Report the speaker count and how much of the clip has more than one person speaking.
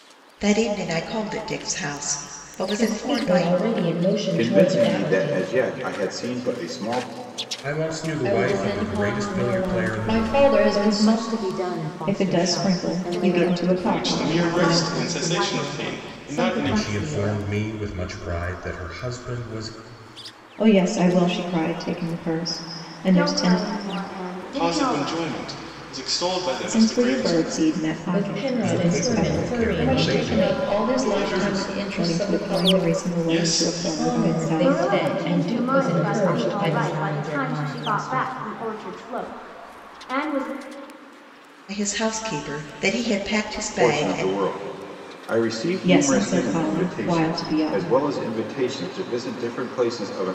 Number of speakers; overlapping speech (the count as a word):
nine, about 51%